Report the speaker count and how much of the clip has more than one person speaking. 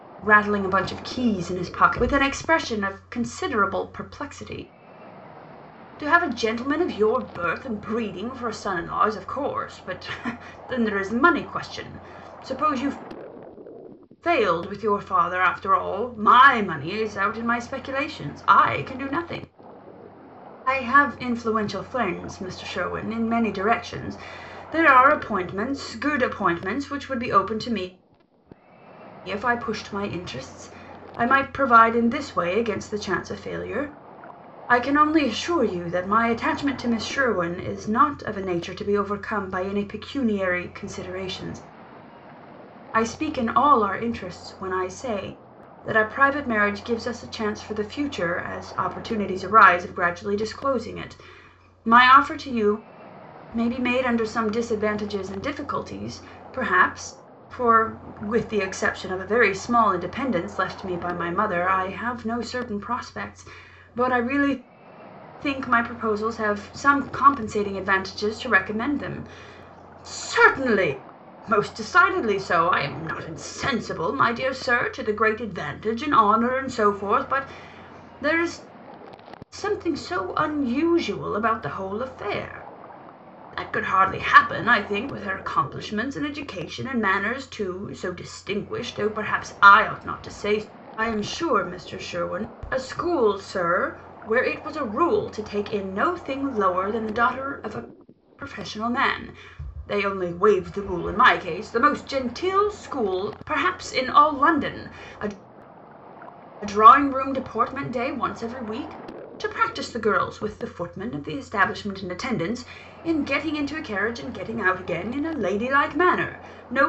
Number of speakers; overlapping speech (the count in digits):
1, no overlap